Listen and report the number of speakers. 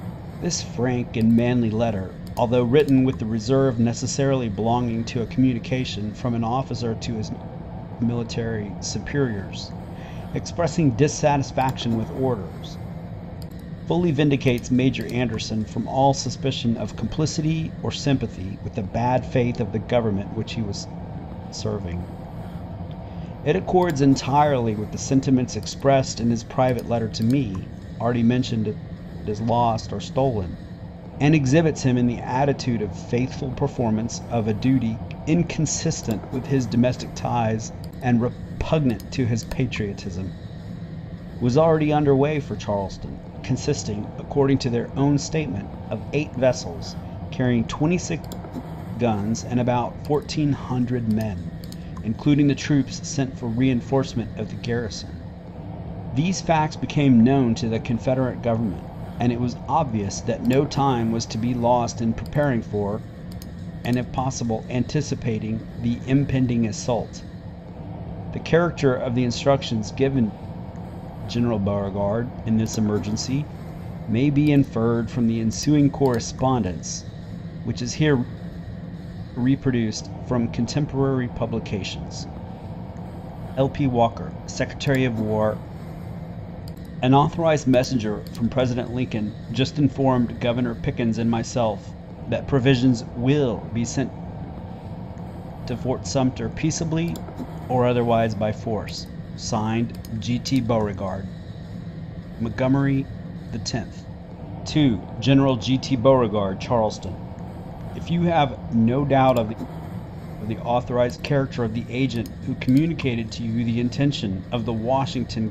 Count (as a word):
one